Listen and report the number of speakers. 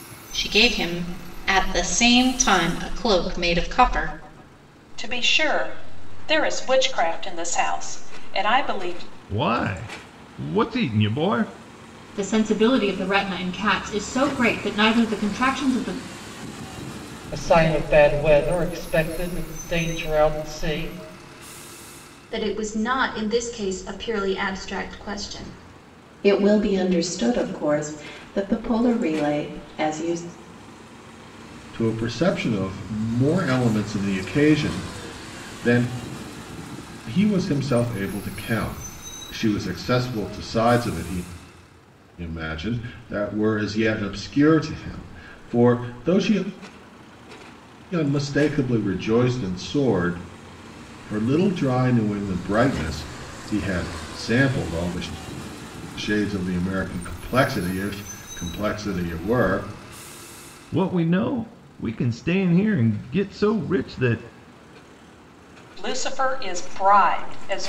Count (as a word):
eight